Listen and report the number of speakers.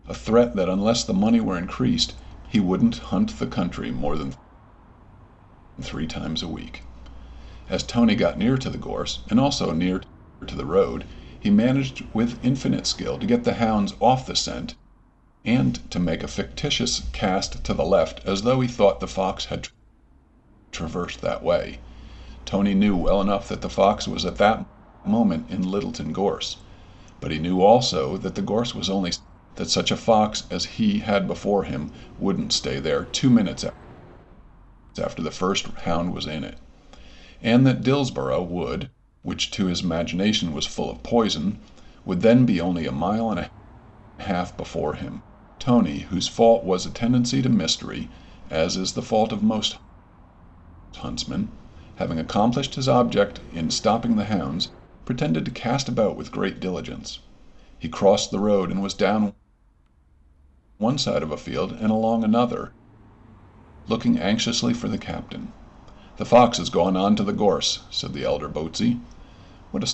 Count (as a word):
one